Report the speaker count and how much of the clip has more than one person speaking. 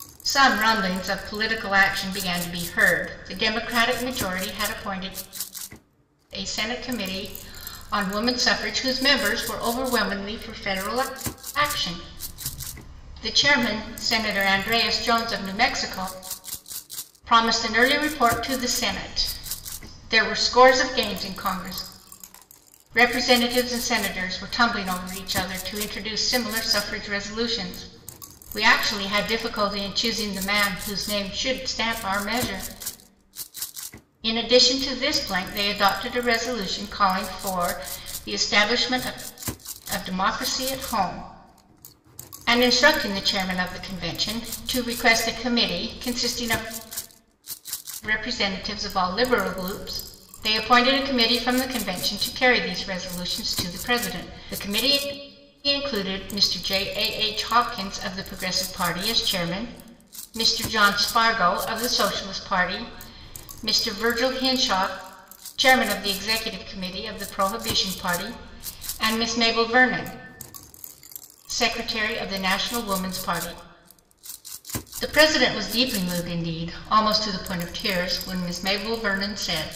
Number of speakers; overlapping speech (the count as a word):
one, no overlap